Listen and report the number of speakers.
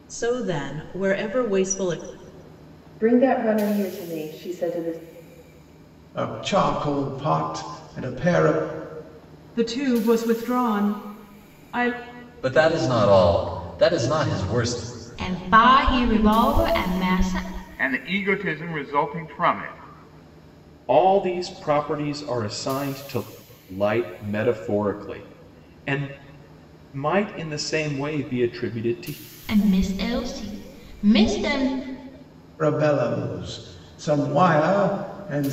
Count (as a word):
eight